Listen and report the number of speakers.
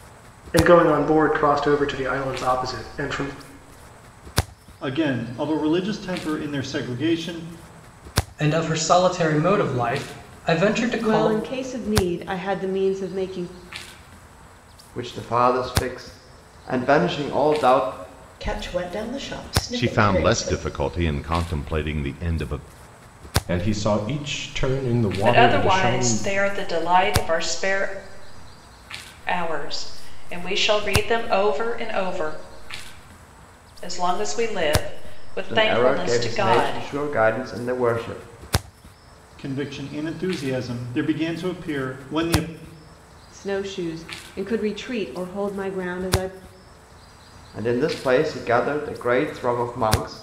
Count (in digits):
9